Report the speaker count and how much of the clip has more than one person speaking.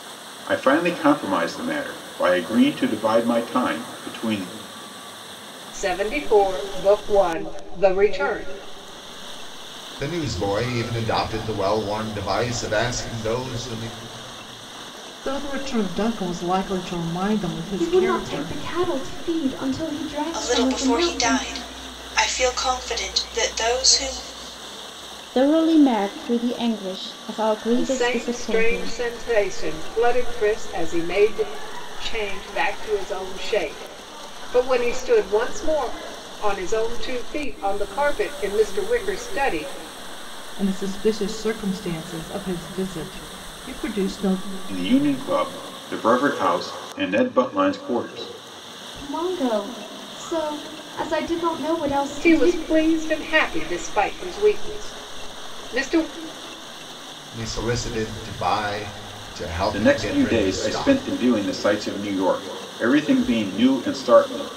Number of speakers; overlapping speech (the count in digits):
7, about 8%